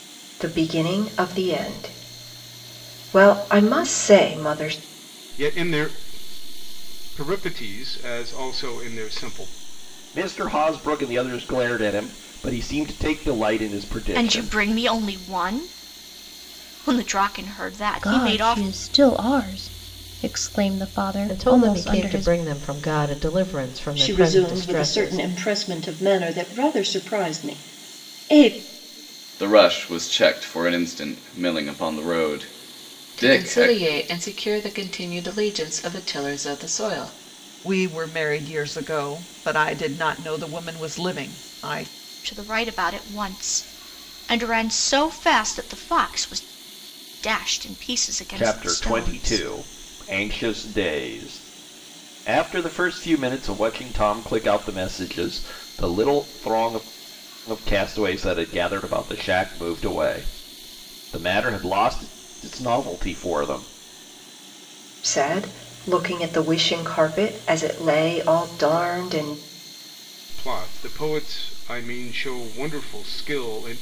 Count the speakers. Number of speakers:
10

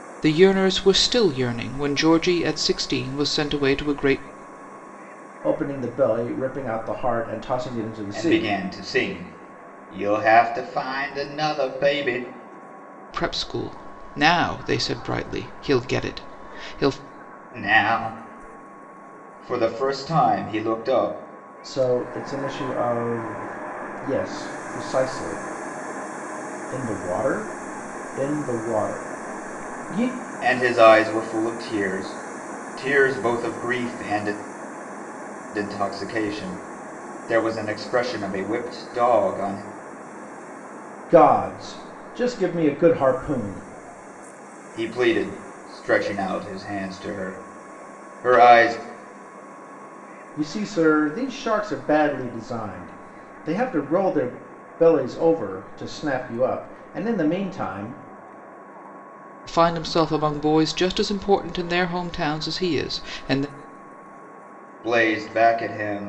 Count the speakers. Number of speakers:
3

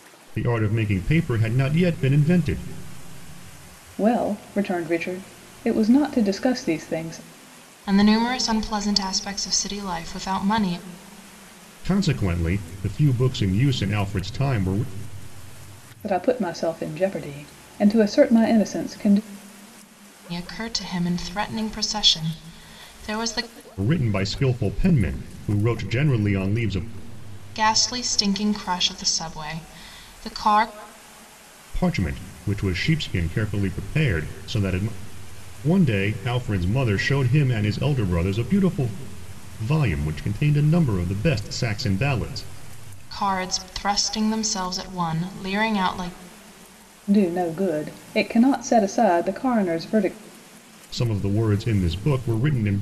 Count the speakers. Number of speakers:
3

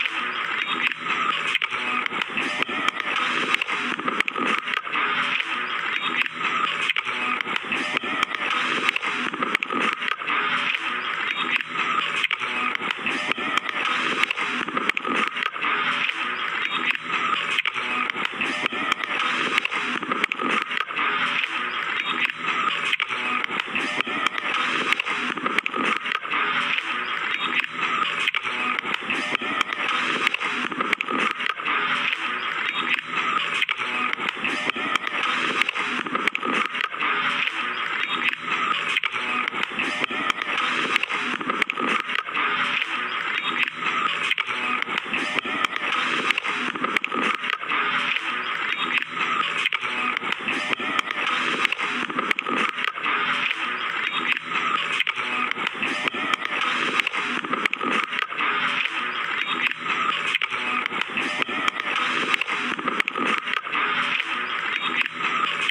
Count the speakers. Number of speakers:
0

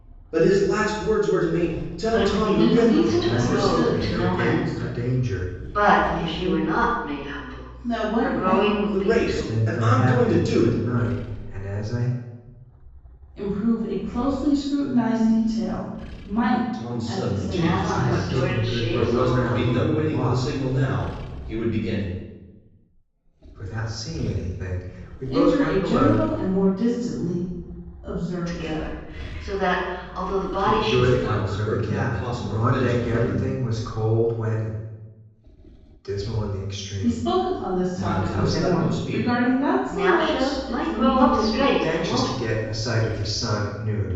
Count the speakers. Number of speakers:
4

